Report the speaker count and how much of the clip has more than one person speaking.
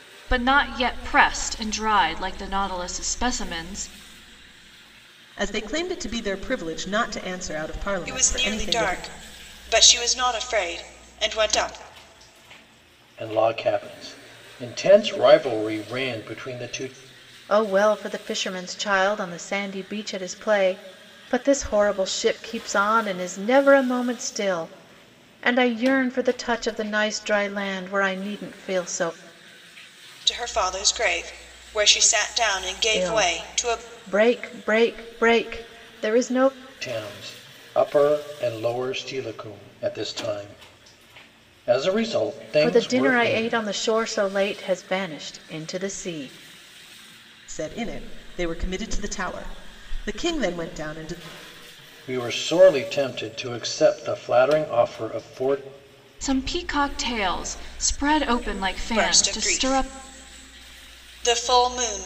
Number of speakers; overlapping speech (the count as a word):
five, about 7%